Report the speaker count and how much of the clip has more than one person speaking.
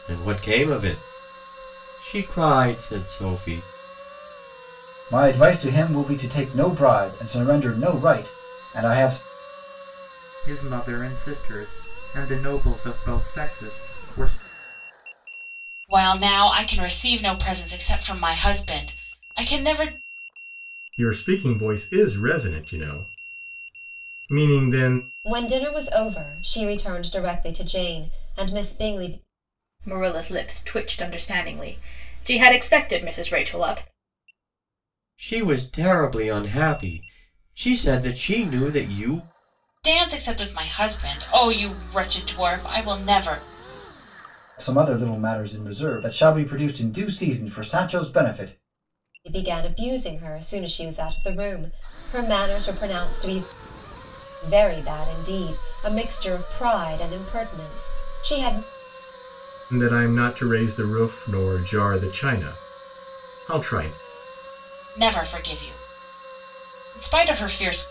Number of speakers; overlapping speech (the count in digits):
7, no overlap